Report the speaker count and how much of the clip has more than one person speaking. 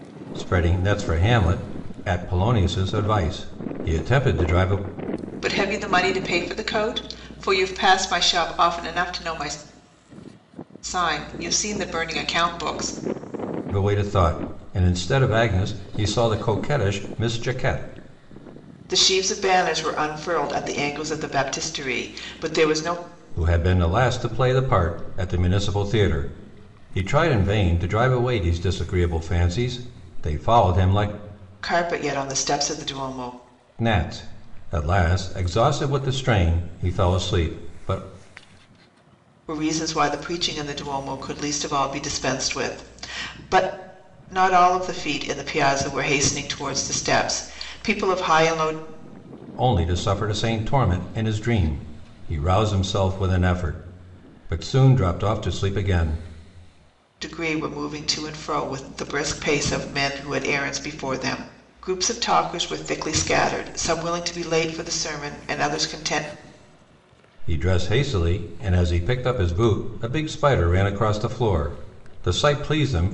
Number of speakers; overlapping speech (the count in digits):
2, no overlap